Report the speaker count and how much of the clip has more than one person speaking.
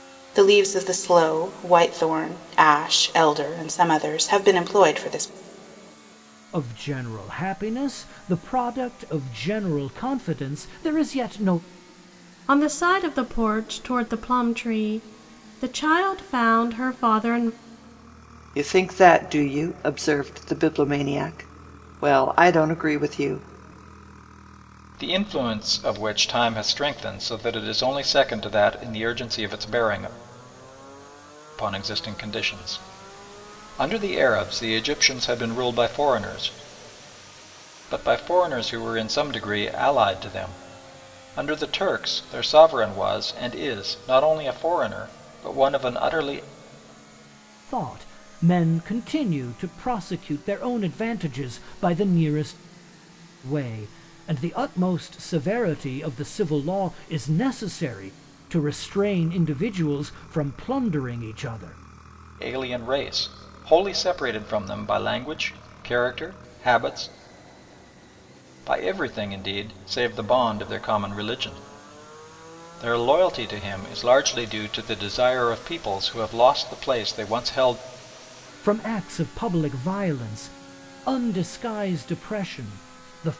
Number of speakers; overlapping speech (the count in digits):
5, no overlap